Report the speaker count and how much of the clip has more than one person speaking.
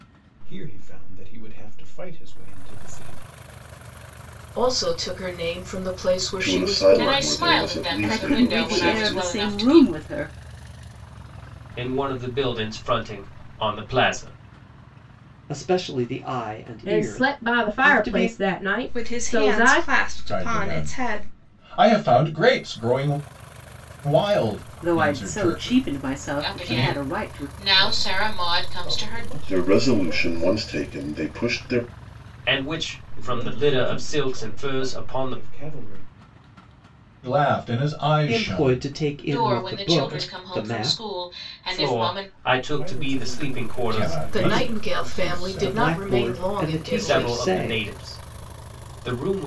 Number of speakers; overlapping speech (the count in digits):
10, about 48%